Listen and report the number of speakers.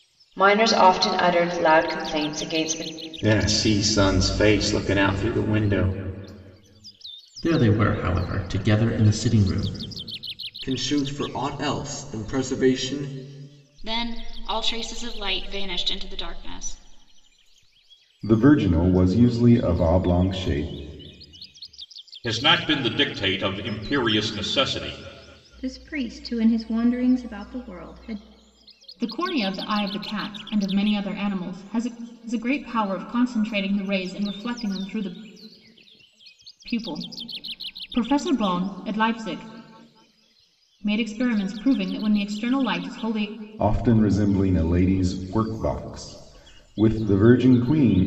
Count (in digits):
9